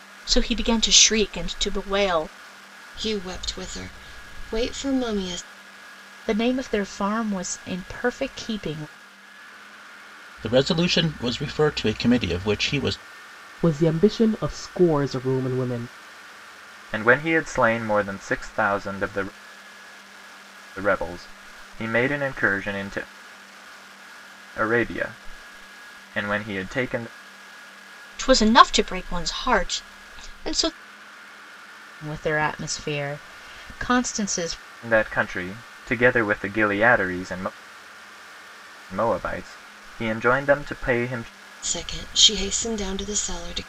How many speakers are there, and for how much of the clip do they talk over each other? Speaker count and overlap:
six, no overlap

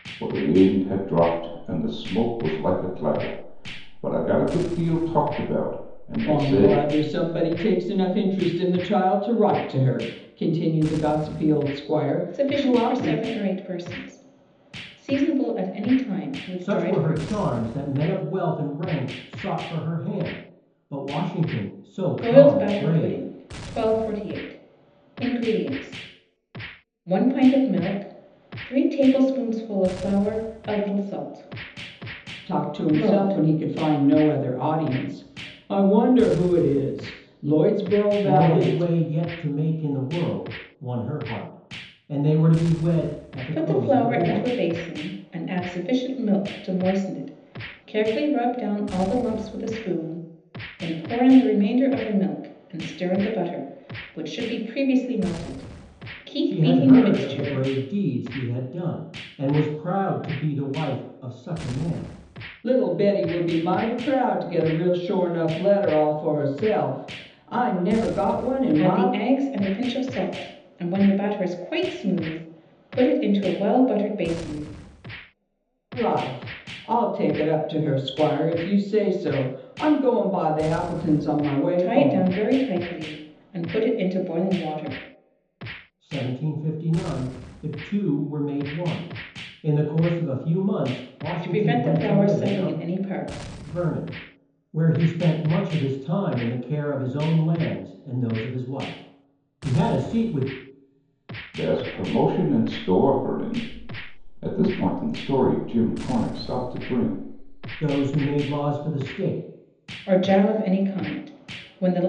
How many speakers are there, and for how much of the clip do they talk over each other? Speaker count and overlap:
four, about 9%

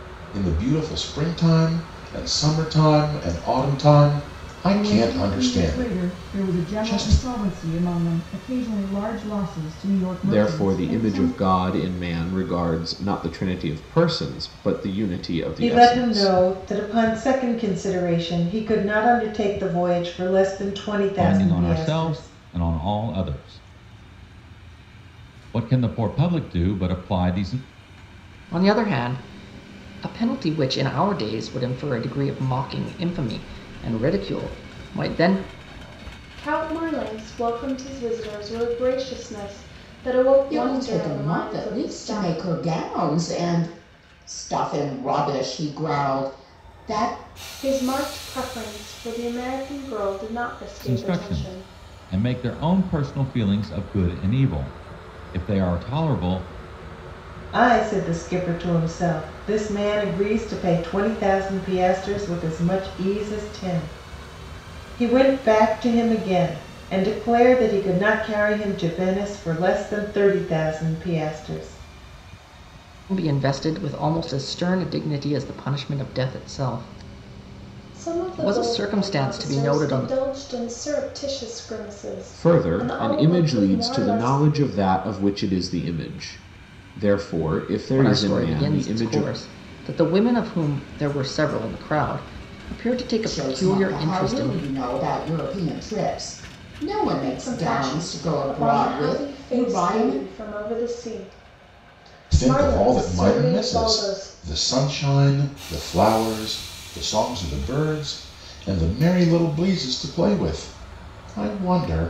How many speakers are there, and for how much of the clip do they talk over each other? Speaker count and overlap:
eight, about 18%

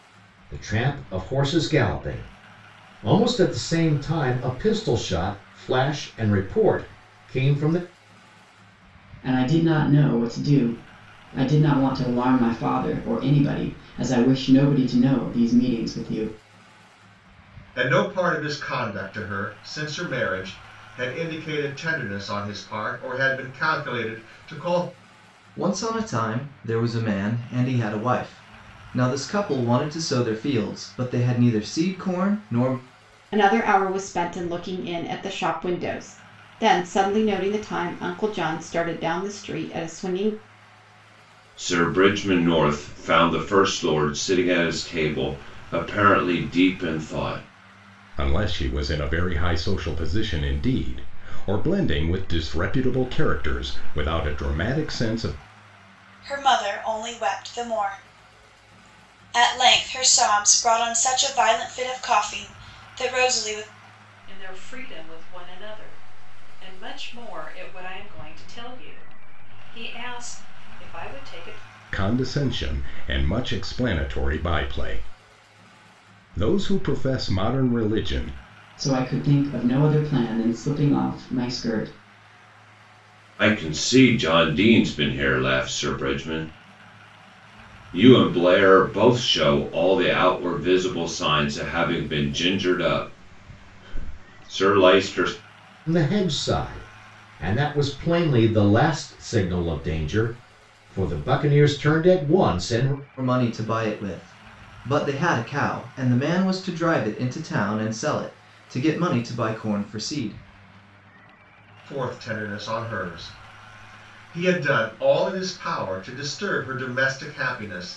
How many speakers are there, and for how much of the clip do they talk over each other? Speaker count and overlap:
nine, no overlap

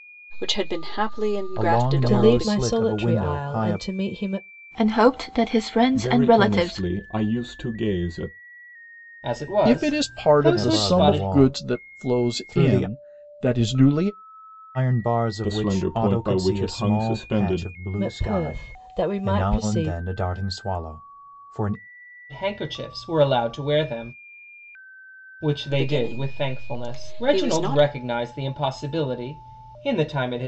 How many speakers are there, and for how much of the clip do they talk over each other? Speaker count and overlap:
seven, about 43%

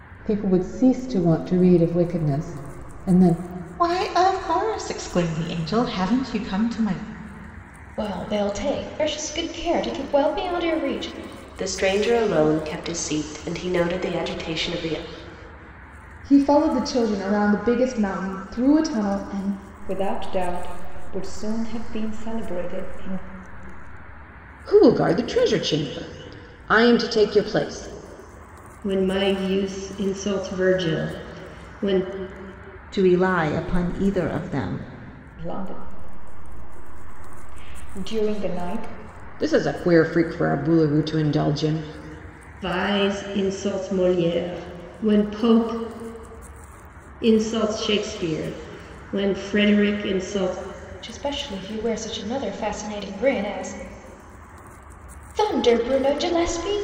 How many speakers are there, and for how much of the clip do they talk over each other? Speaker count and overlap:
nine, no overlap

